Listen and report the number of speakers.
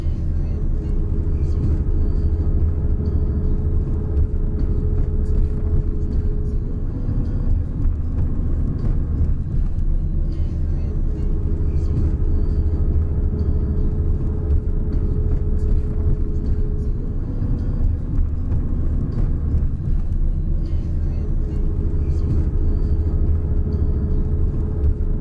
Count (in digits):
0